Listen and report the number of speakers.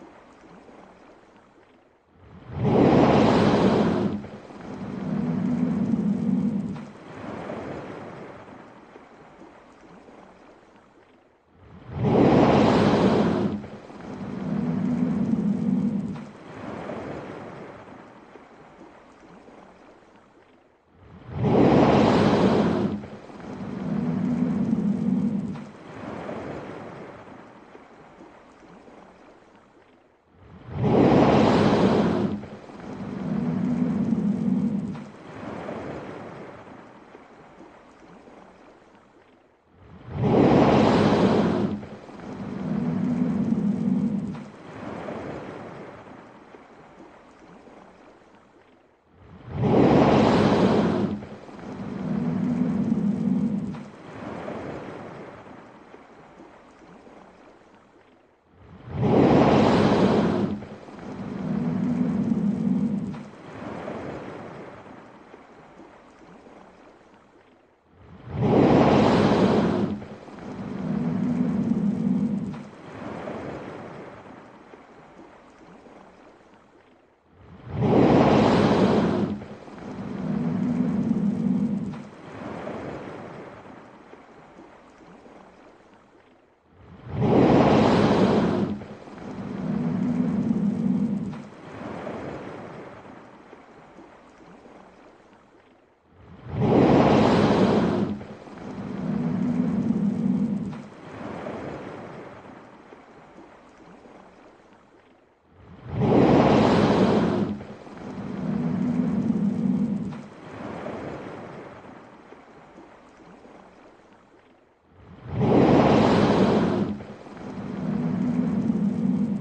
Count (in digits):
0